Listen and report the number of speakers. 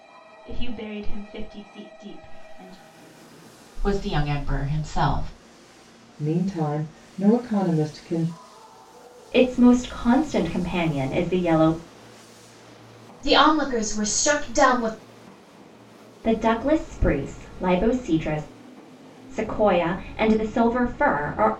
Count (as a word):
five